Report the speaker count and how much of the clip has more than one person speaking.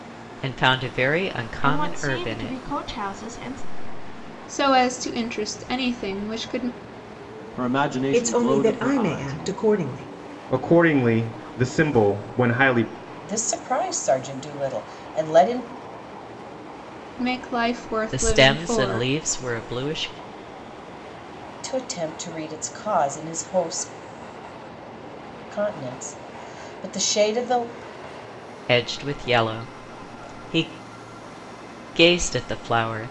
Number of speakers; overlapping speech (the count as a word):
seven, about 11%